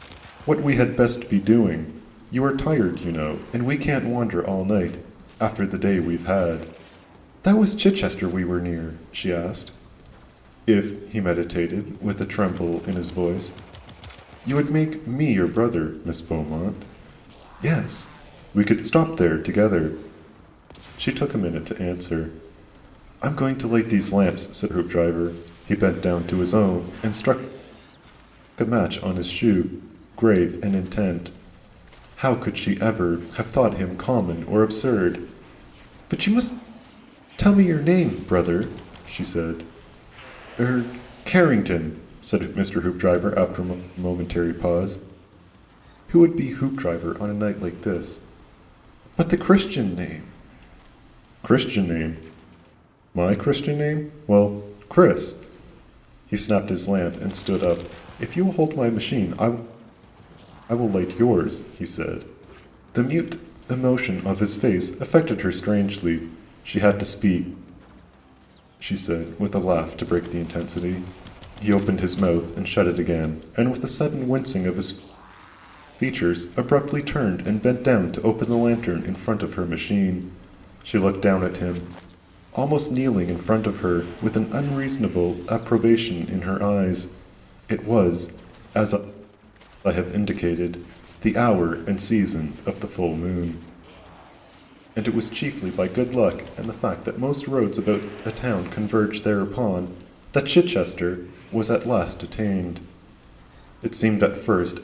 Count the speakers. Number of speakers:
one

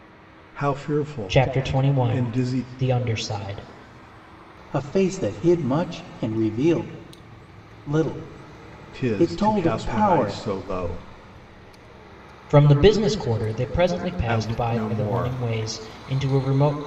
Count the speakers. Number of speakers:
three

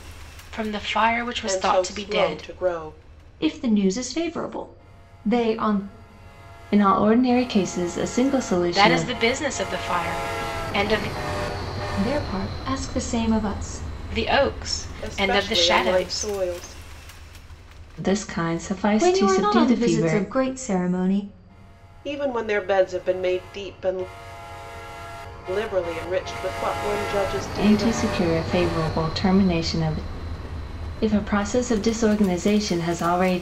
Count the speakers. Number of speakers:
four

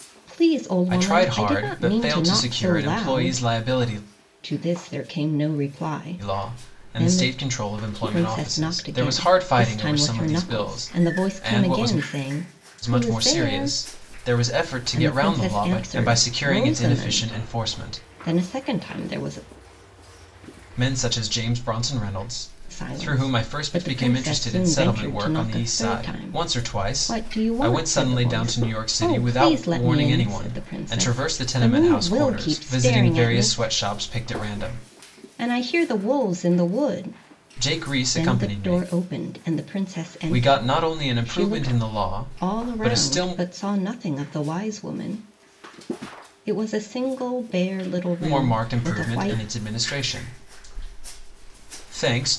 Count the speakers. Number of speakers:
two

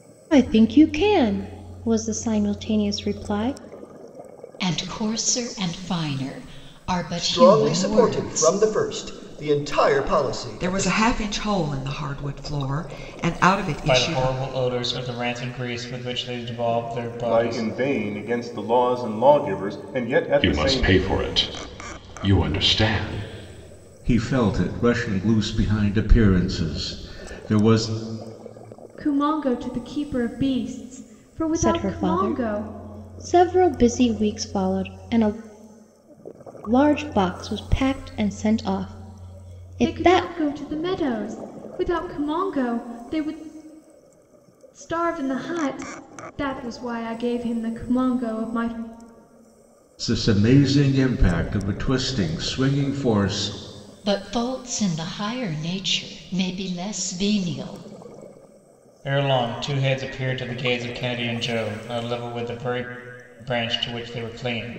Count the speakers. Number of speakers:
nine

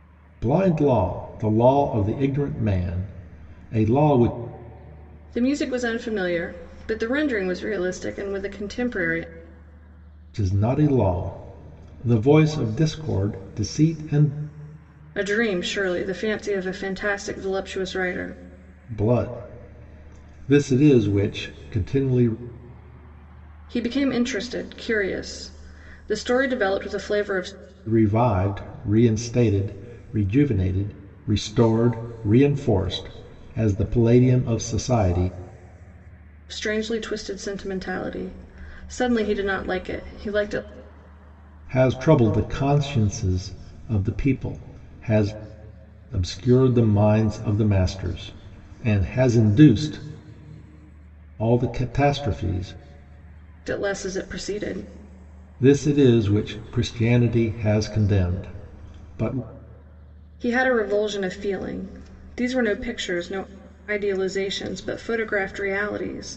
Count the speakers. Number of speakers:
two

